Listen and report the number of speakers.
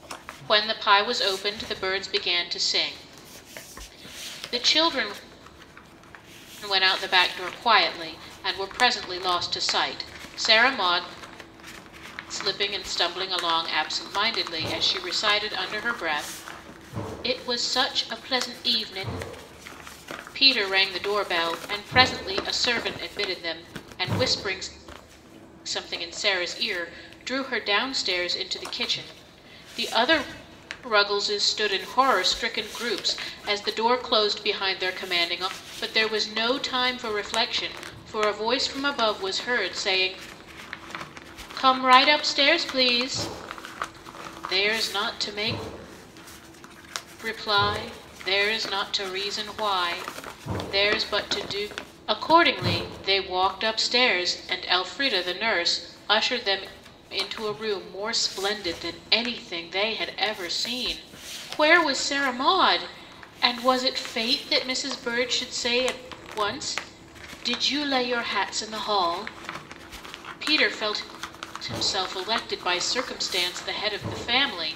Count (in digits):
1